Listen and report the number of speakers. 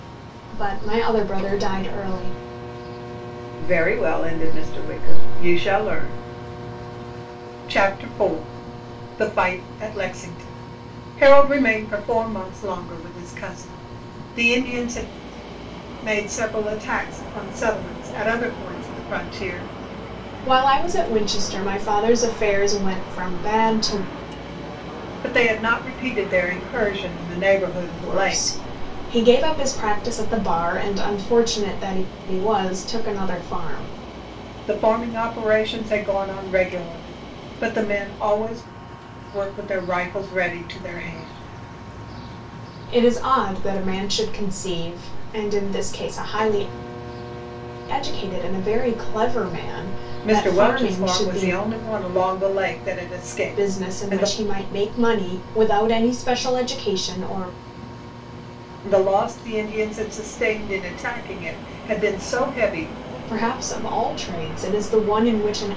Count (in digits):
2